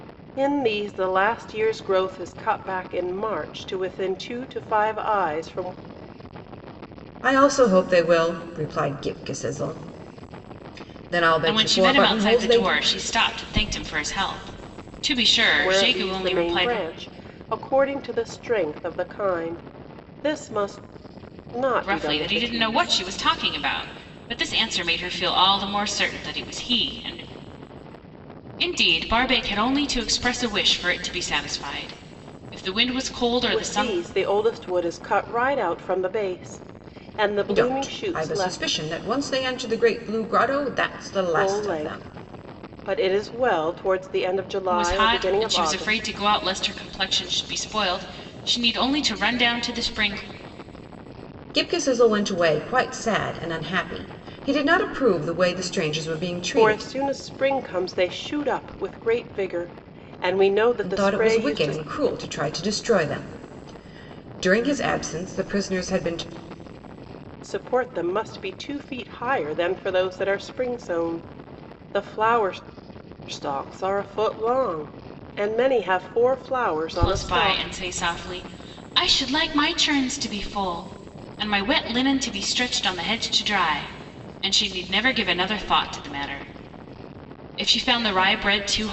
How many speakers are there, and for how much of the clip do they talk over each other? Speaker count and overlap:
three, about 11%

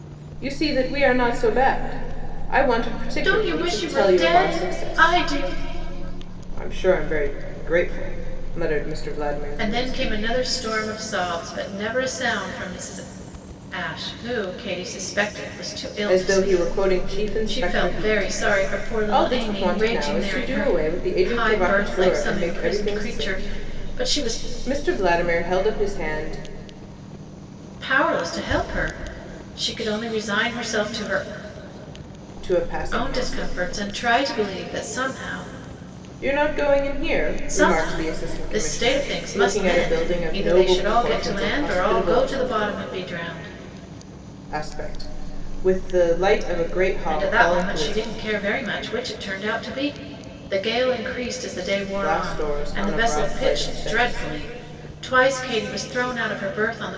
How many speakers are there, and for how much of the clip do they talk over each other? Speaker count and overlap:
two, about 33%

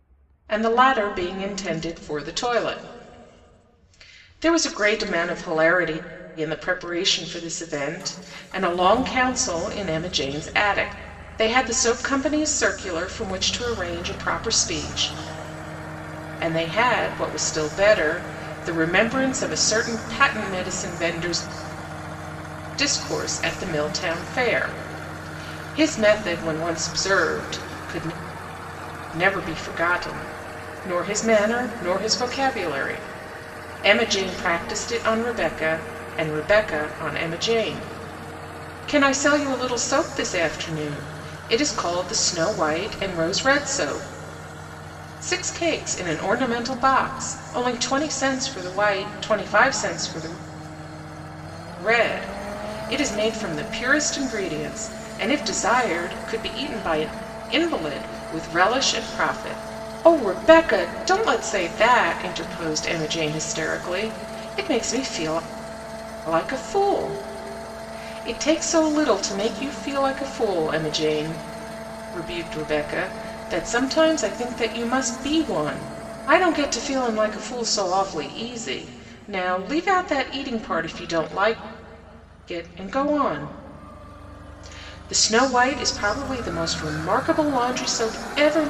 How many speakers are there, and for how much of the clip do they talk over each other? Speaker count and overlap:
one, no overlap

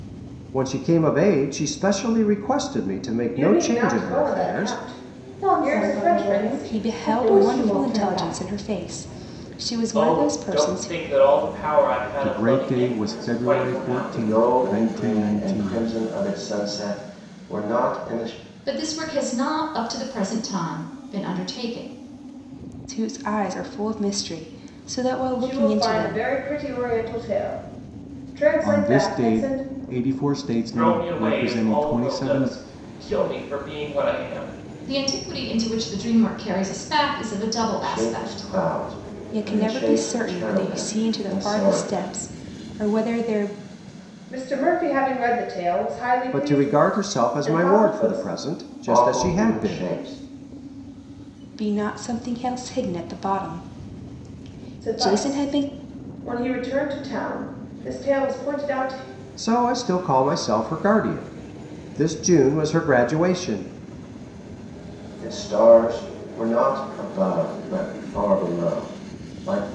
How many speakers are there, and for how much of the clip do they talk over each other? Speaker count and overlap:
eight, about 30%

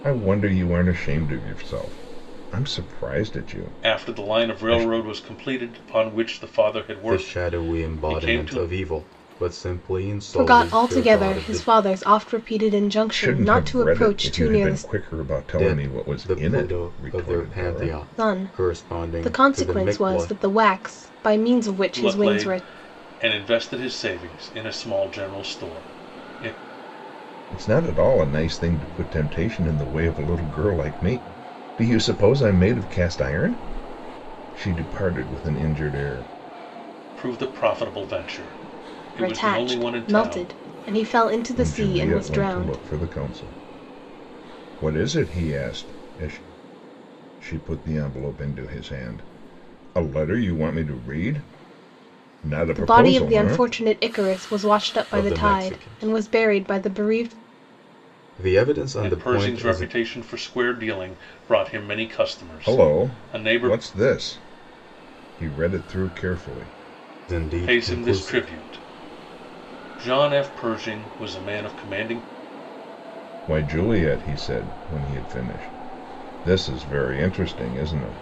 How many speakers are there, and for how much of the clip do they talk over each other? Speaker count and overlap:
four, about 26%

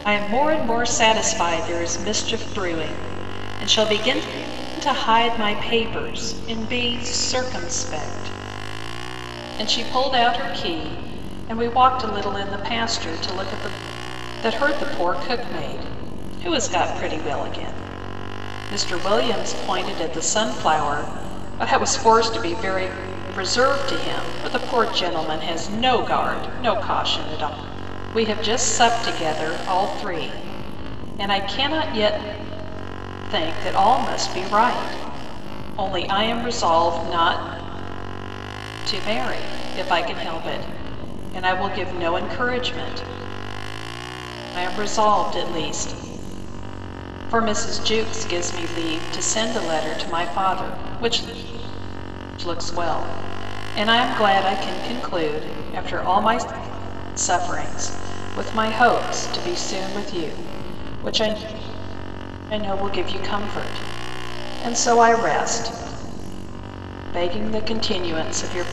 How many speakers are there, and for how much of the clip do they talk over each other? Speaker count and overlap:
one, no overlap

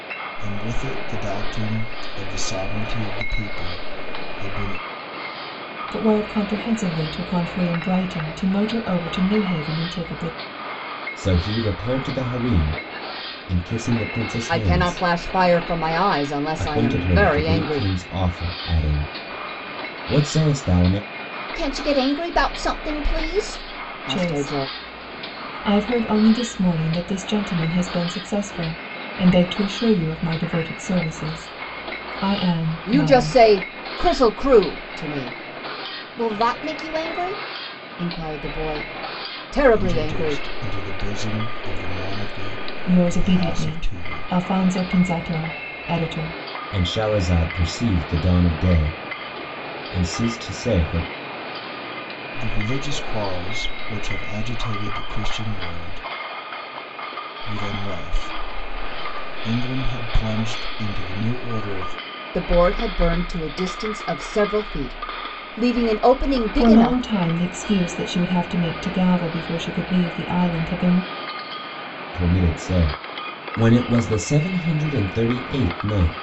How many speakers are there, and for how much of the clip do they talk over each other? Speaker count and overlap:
four, about 8%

